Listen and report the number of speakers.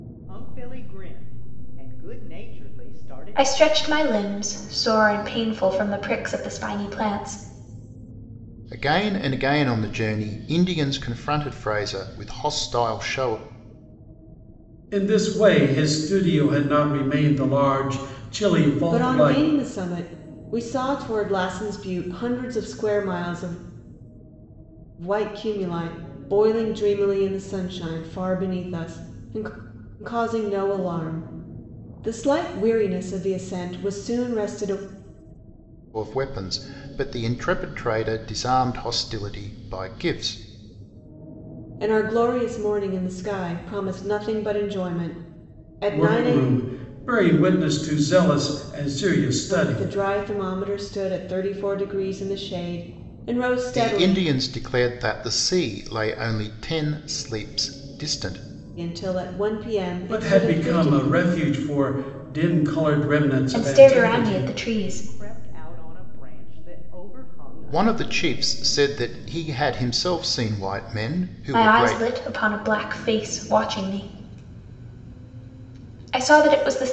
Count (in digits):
5